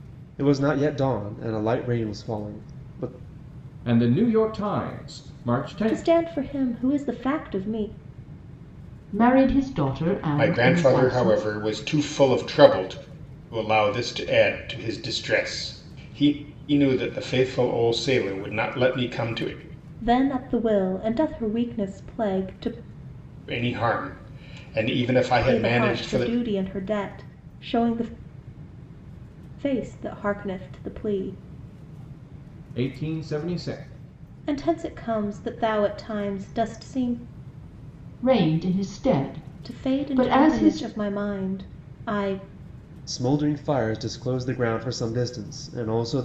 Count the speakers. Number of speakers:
5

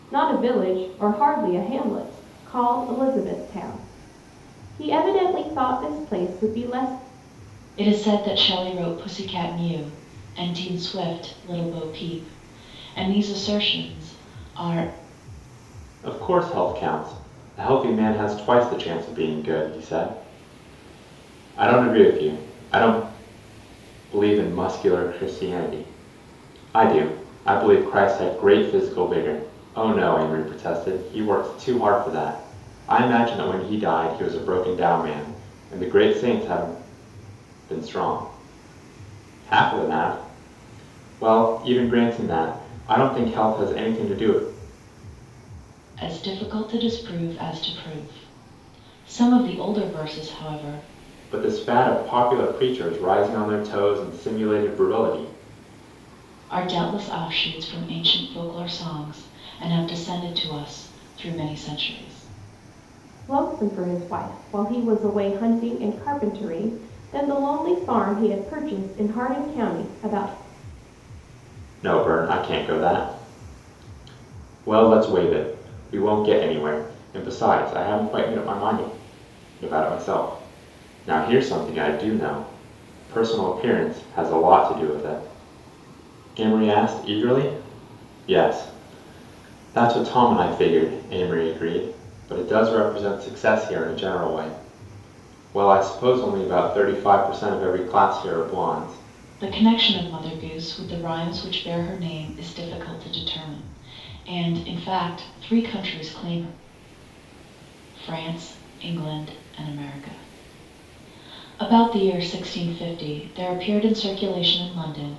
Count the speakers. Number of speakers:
3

